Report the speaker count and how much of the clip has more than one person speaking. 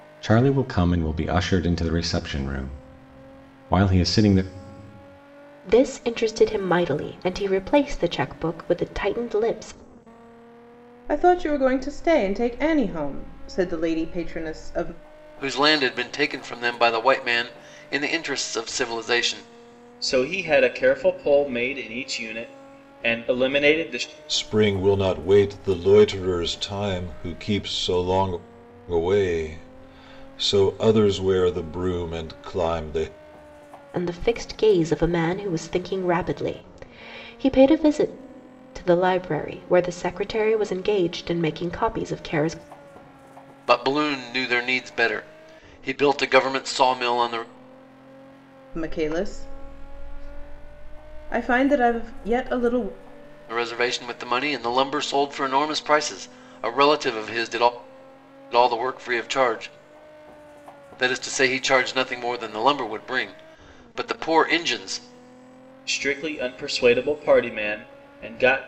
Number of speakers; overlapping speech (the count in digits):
6, no overlap